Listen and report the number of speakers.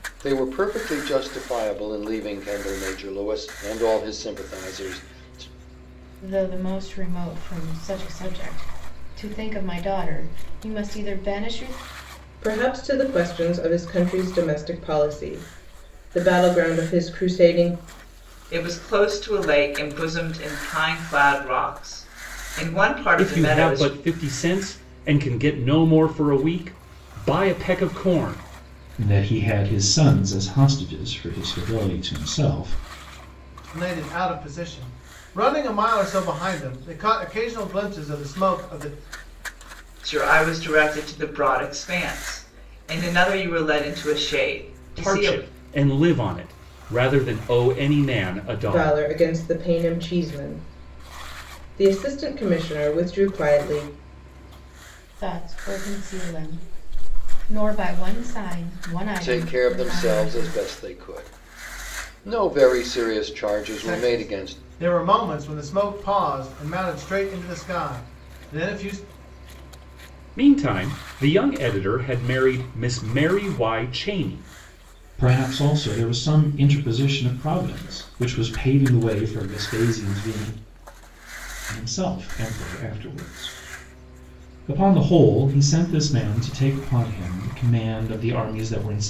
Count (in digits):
7